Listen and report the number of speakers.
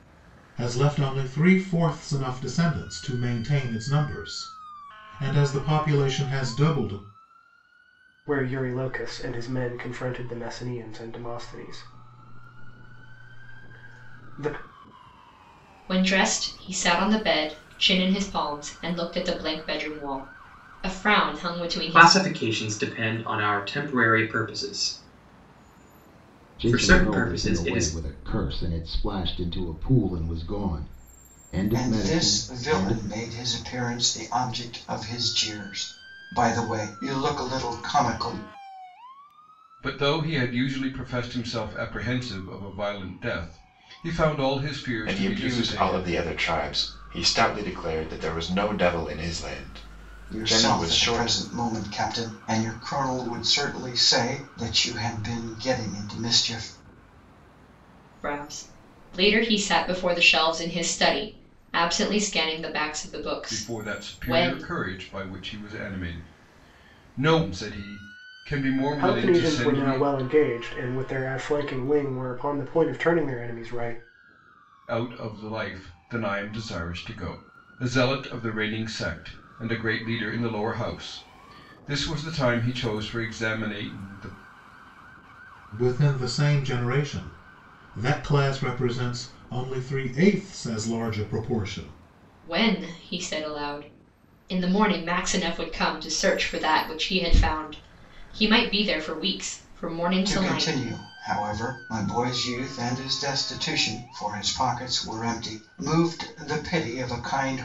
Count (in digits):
8